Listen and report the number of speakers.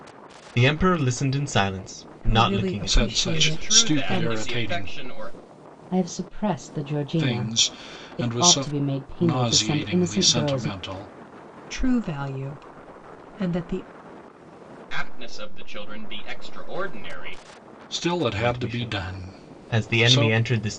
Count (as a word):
five